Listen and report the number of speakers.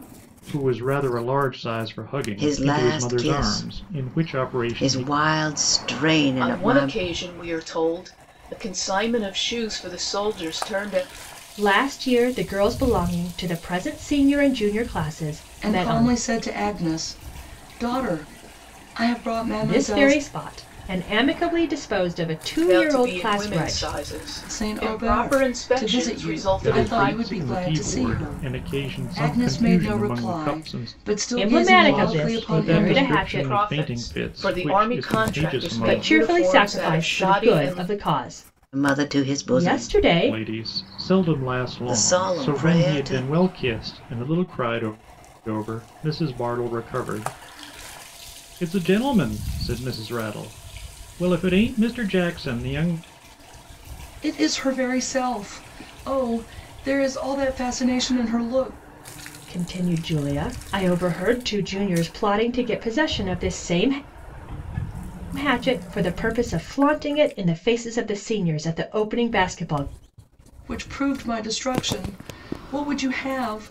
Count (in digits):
5